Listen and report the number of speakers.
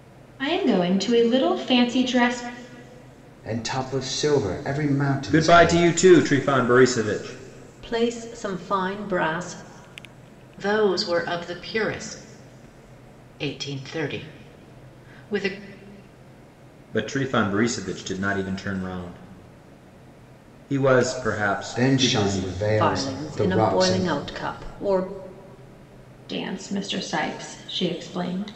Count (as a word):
five